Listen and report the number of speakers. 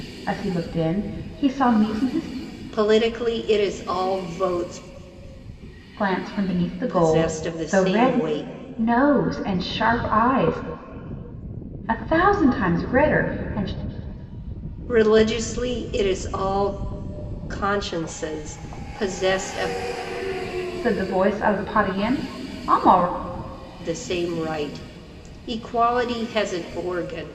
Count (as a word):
two